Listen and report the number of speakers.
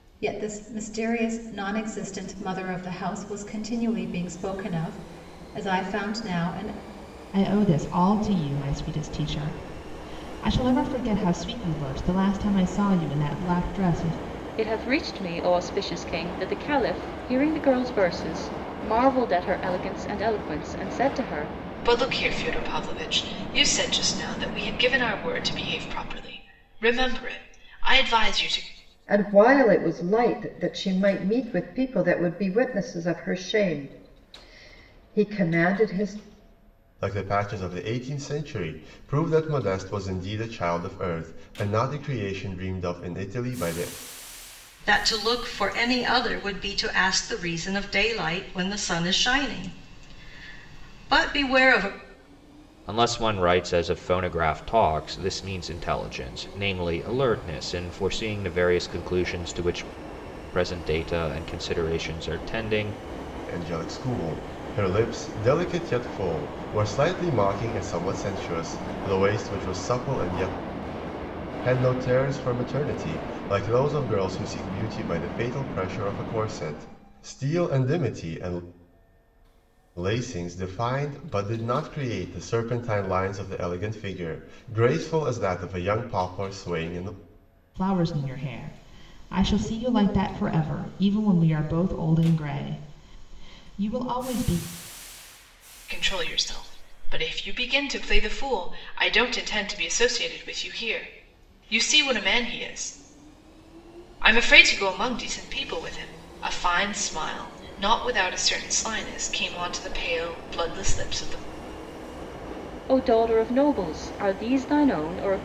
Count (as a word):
eight